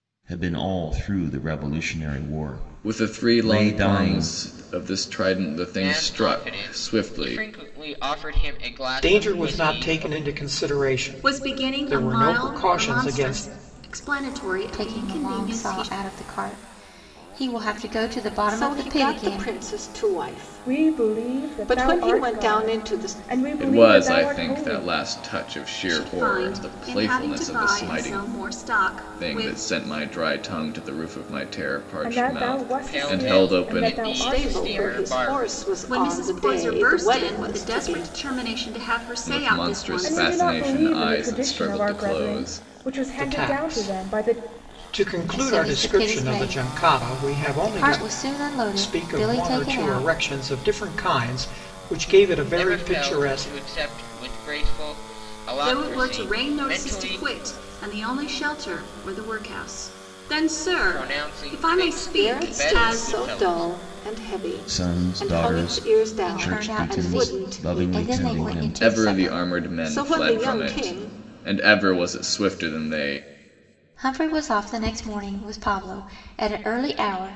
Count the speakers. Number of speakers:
8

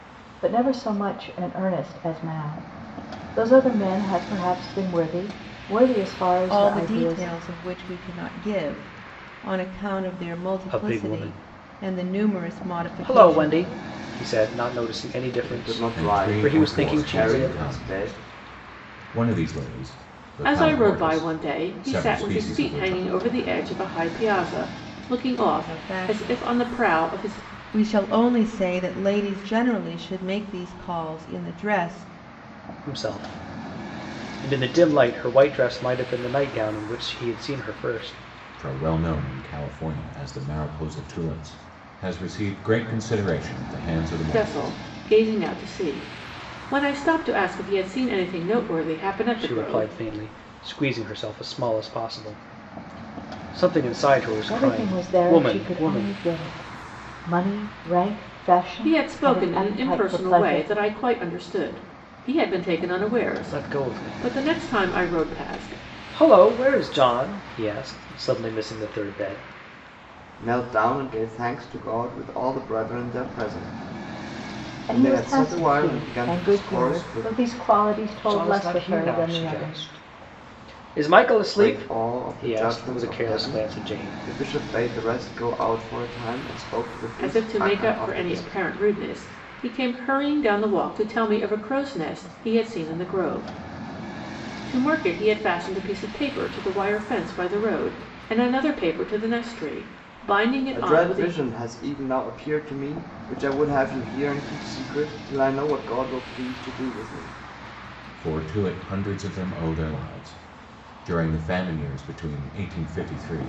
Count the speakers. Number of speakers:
6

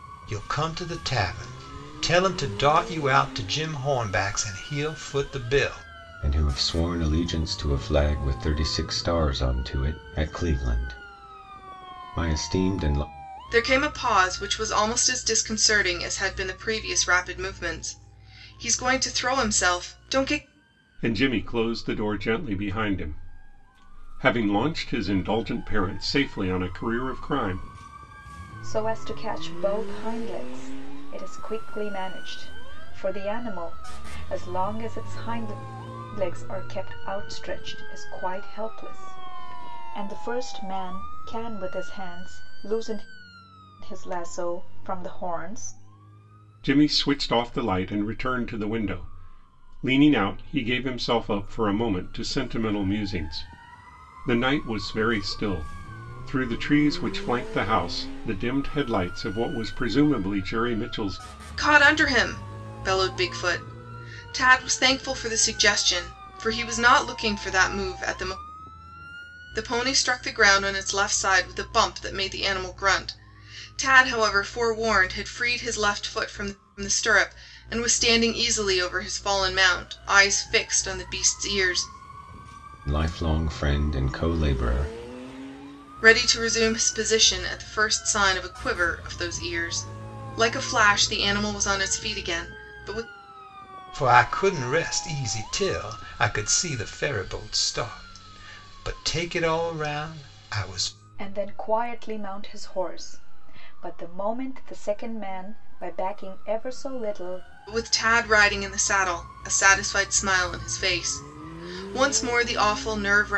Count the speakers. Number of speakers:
5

